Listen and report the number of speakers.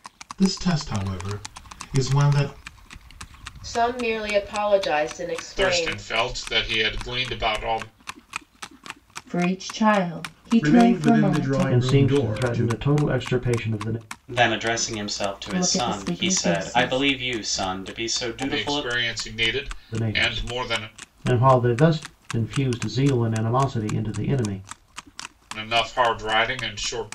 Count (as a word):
seven